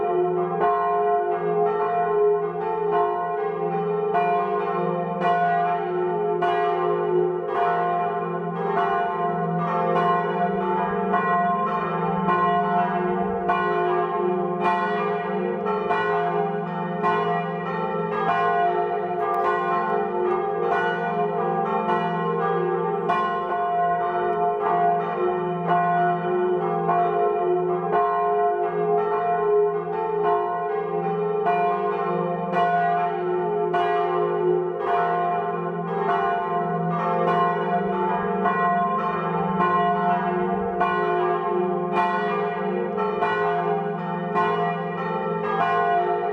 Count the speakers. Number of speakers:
0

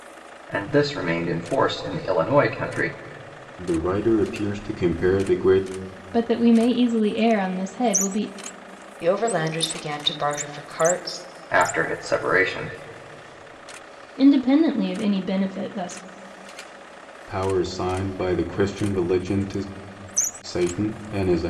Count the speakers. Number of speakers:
4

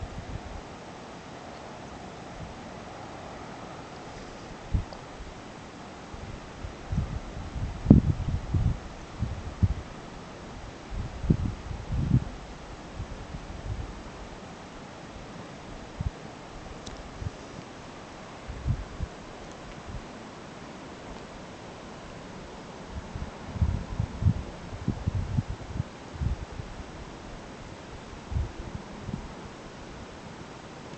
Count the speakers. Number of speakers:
0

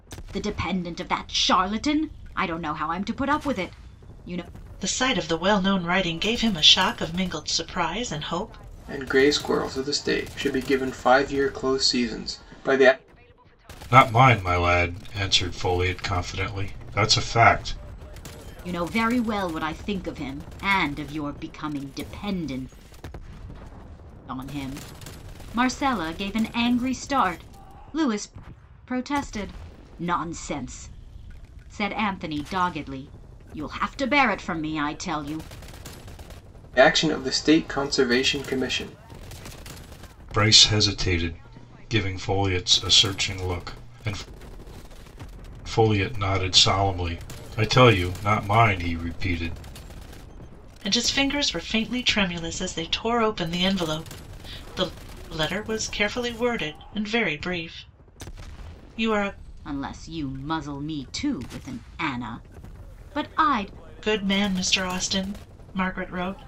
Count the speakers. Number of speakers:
4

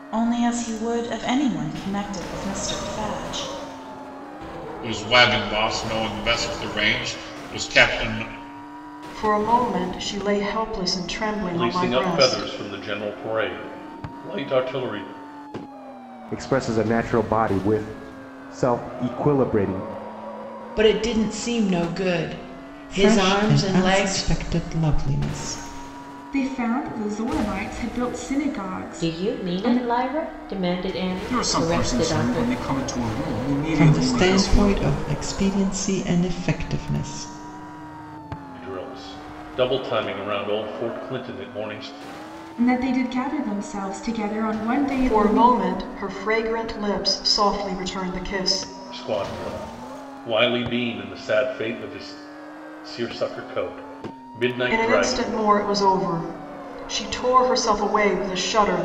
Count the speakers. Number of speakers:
10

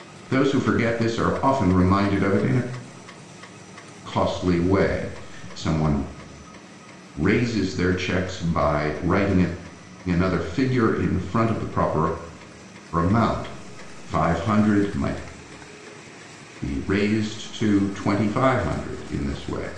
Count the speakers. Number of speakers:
1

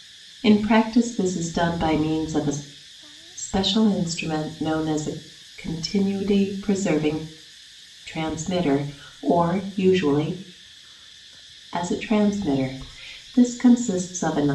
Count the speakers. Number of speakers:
1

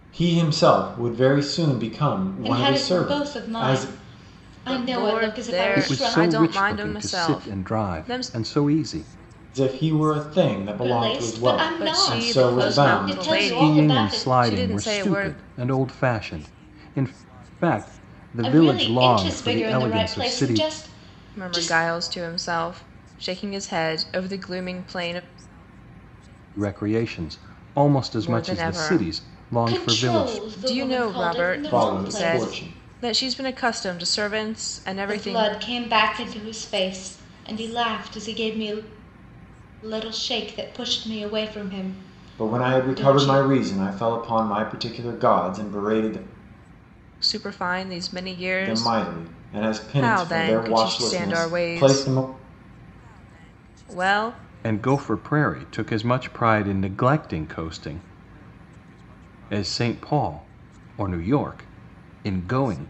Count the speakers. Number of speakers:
4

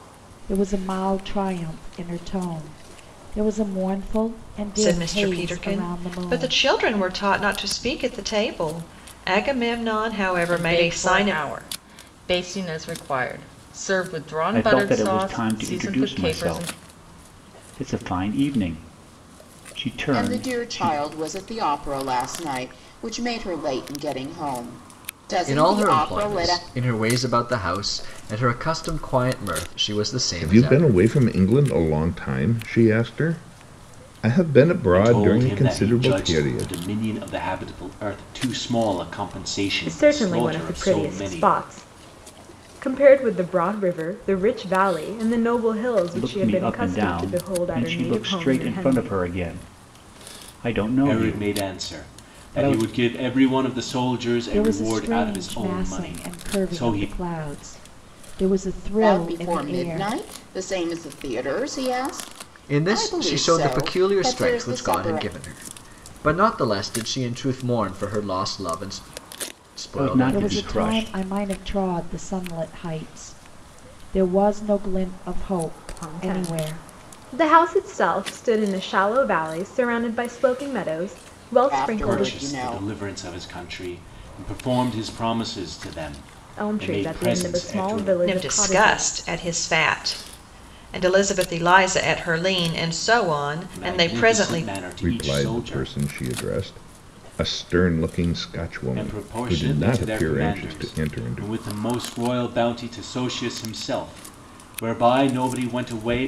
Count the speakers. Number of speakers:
9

